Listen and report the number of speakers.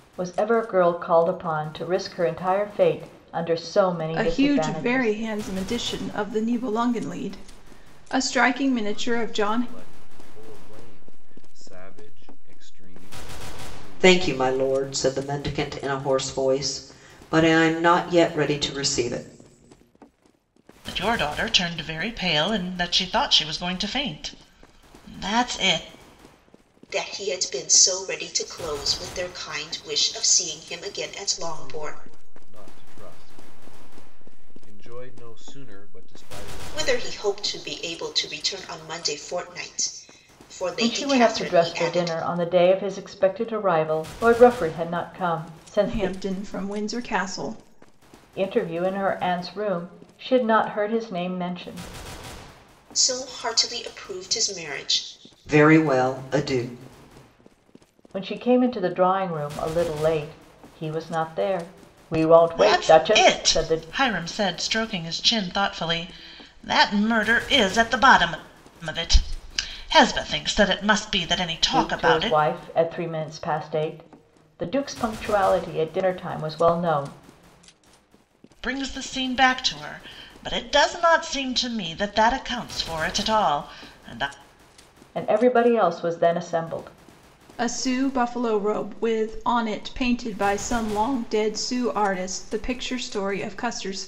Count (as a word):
six